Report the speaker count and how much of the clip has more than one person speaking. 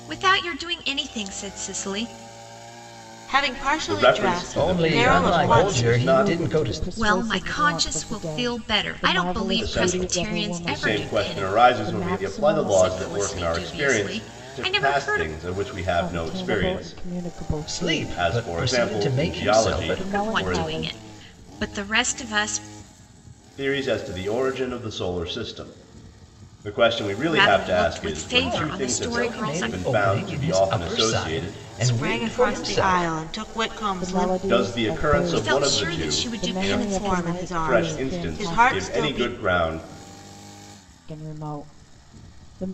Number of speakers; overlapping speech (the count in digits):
5, about 63%